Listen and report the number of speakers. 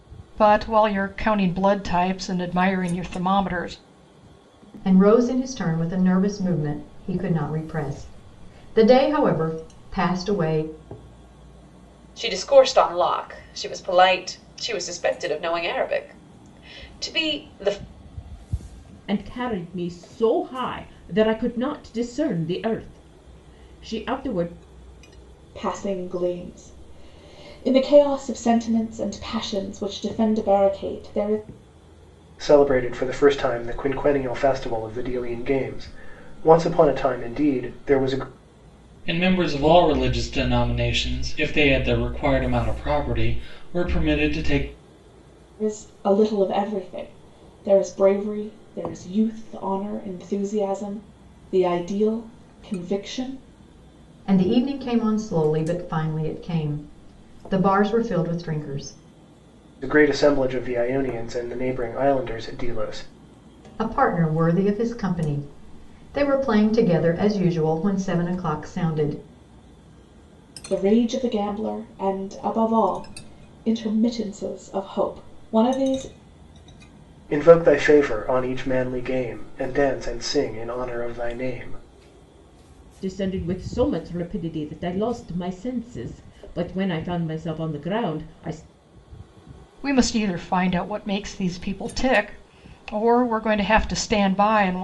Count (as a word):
seven